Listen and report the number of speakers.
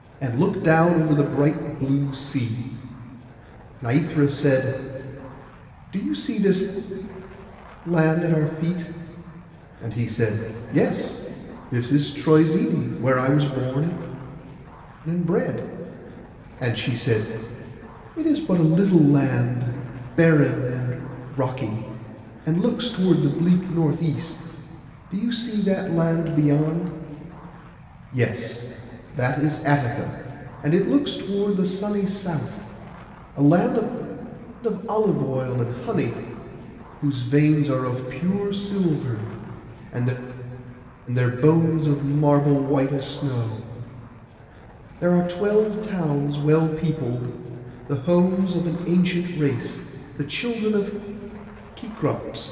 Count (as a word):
one